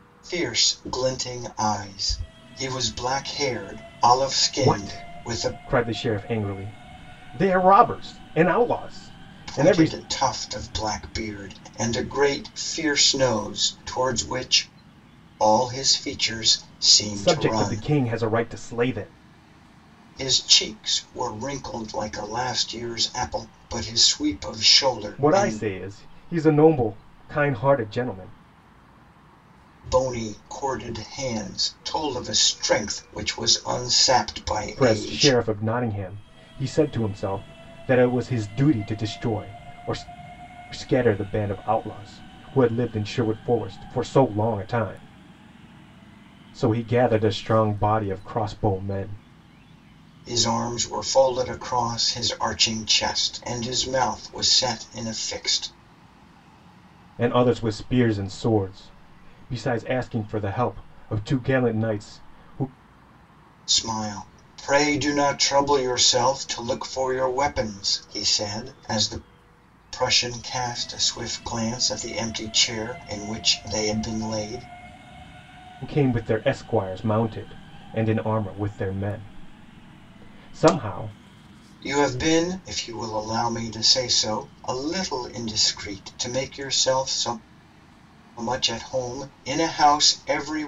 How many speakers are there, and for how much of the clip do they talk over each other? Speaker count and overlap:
two, about 4%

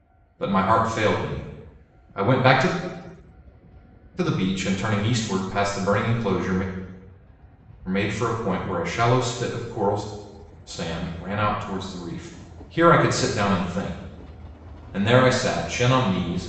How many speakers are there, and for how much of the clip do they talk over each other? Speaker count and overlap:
one, no overlap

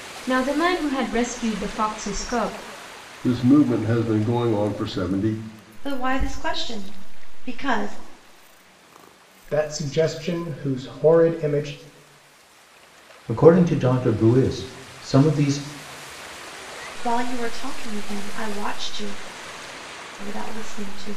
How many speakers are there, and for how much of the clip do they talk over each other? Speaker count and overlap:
five, no overlap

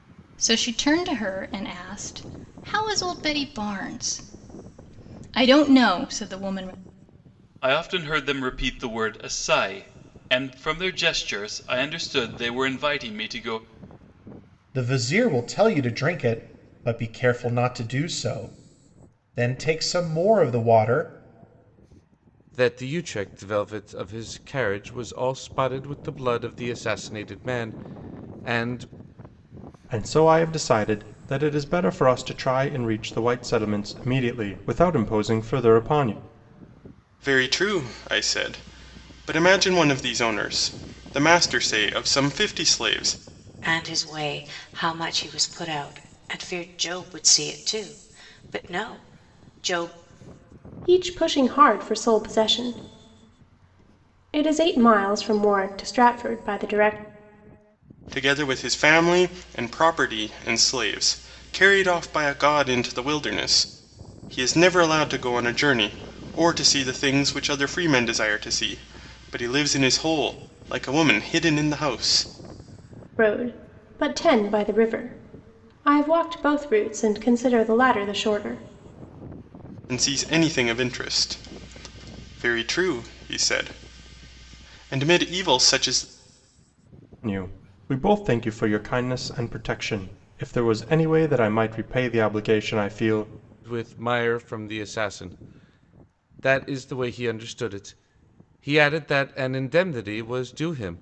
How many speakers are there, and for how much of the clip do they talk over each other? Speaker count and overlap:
eight, no overlap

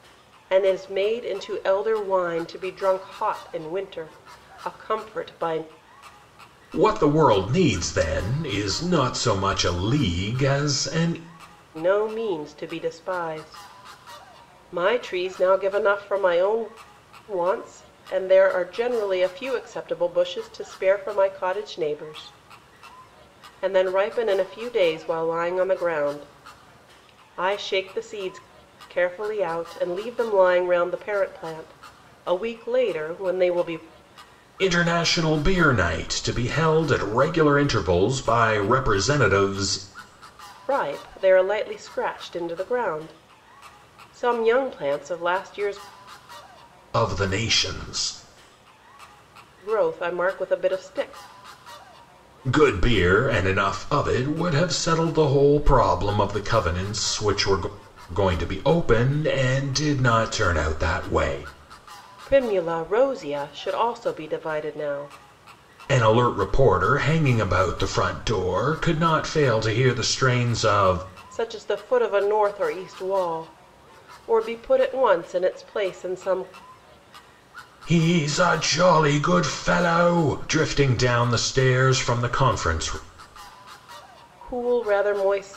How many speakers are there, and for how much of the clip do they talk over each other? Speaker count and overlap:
two, no overlap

